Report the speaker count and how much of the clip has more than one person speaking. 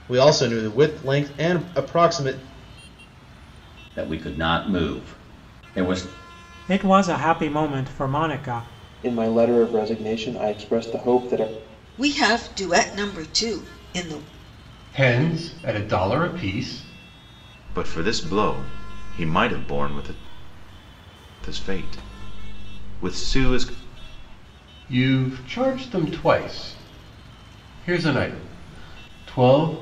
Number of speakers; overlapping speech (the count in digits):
7, no overlap